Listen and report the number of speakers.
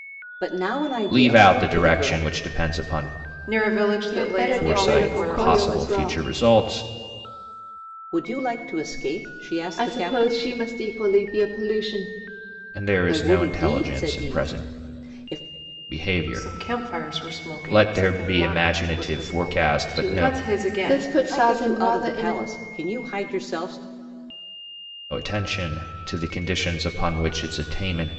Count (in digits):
4